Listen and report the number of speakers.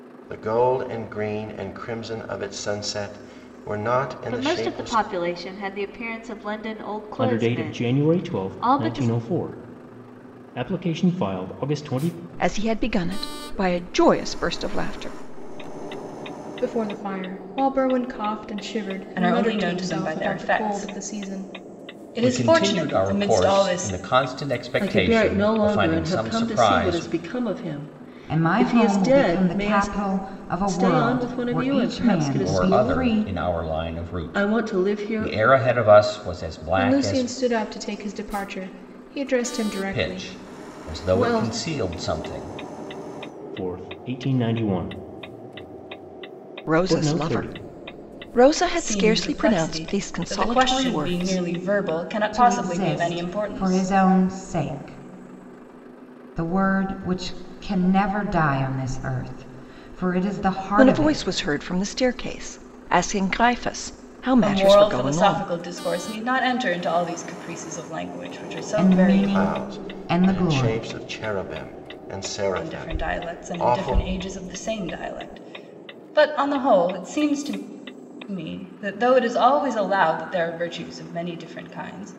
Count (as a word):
nine